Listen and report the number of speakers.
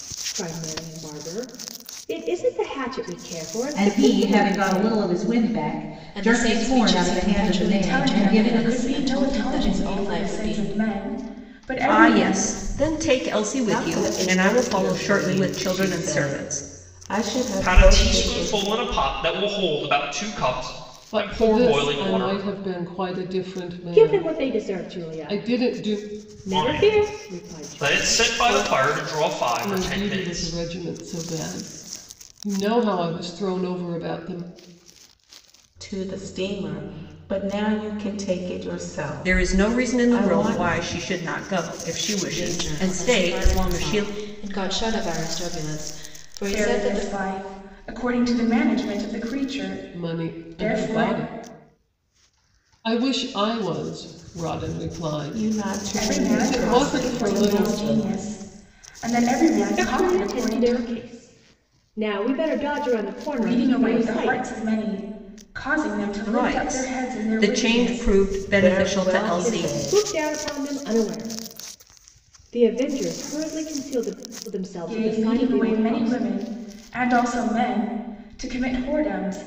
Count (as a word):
eight